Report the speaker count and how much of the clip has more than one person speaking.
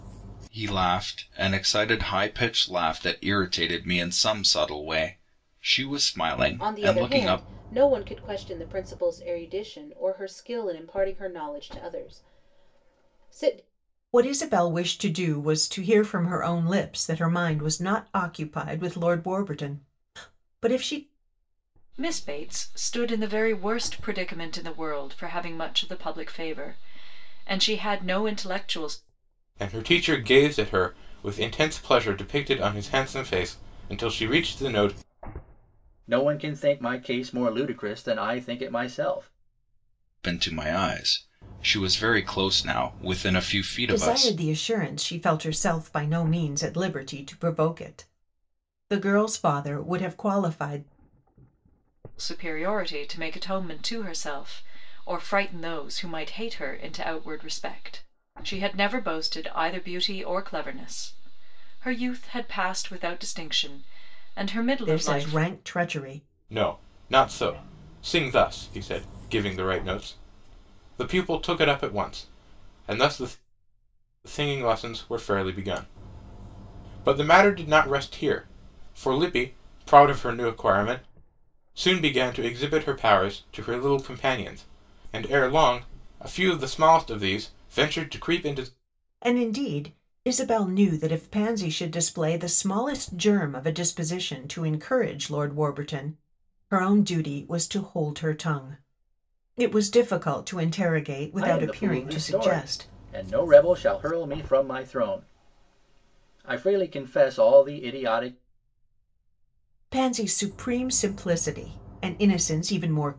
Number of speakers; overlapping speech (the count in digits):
6, about 3%